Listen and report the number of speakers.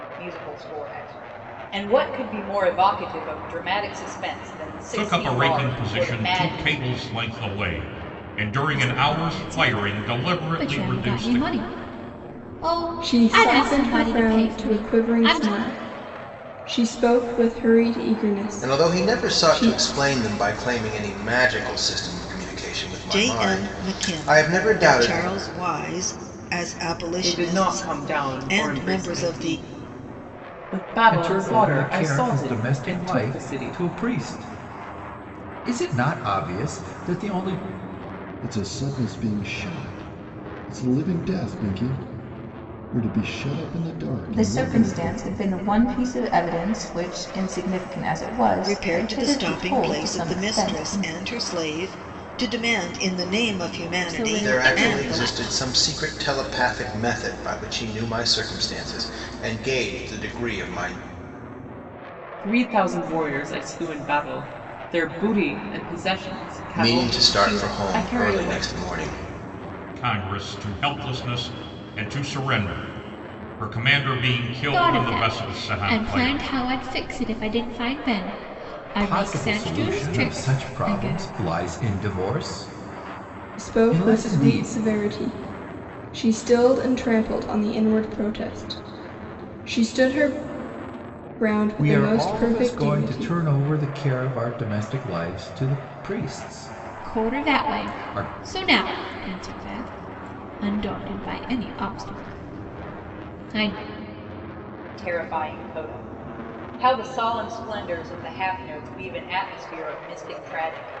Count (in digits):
10